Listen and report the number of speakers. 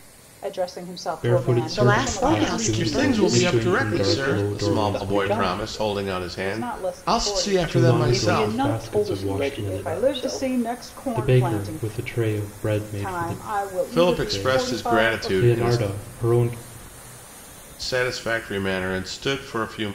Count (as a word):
five